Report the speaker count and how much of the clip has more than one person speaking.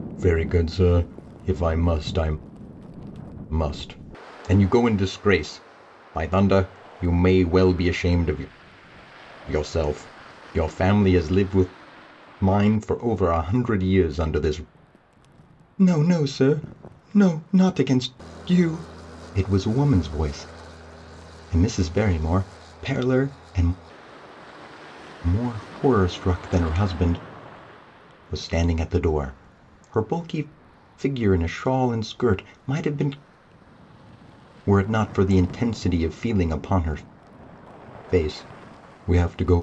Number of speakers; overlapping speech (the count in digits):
1, no overlap